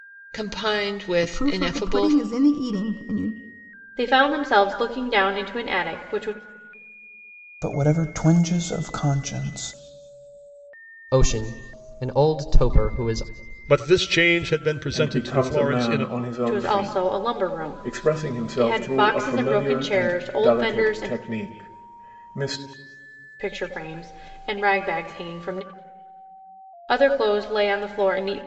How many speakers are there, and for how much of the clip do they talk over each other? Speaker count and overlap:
seven, about 21%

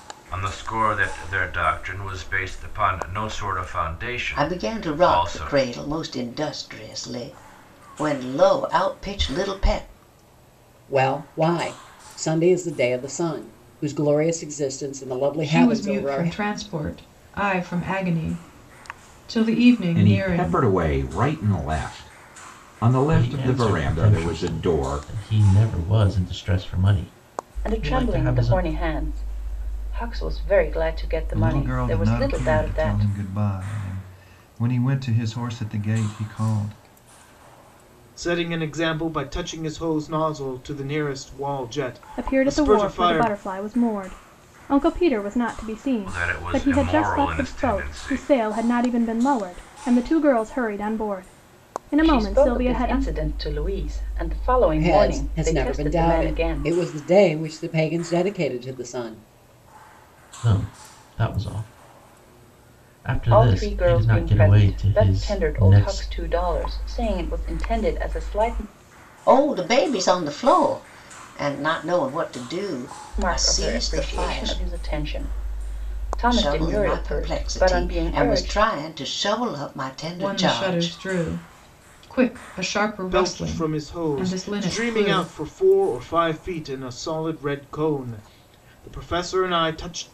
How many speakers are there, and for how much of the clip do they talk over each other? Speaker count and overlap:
ten, about 26%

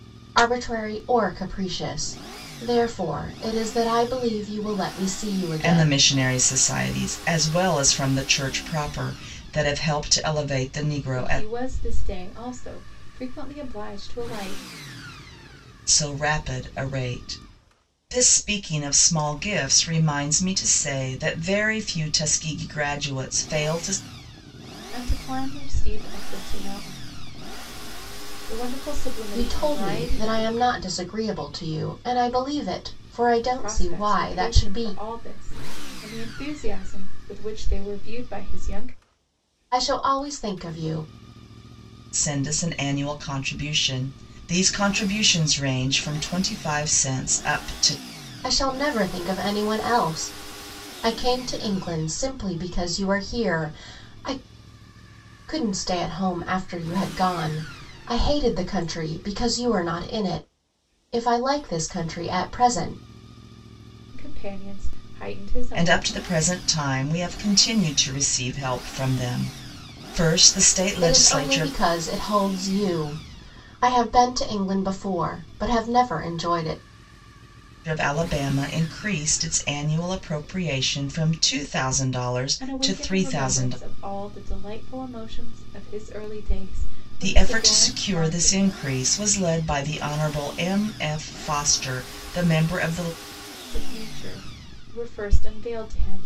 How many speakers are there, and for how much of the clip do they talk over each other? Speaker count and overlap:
three, about 8%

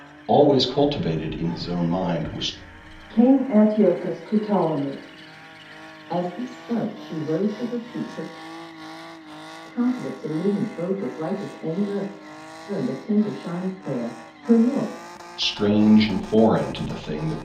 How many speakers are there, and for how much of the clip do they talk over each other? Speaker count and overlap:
three, no overlap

